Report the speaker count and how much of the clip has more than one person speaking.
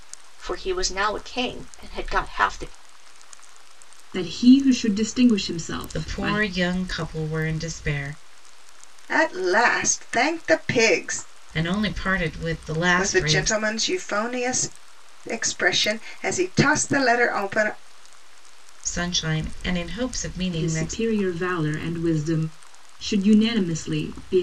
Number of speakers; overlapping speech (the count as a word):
four, about 7%